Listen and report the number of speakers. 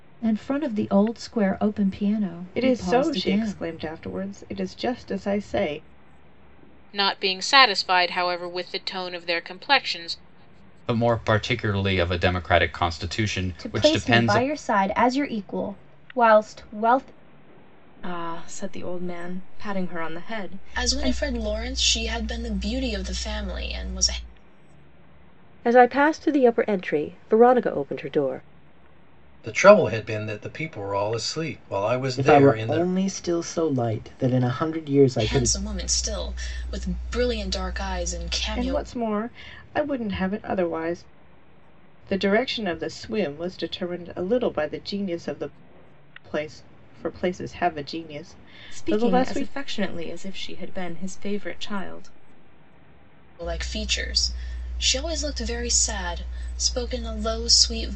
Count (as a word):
ten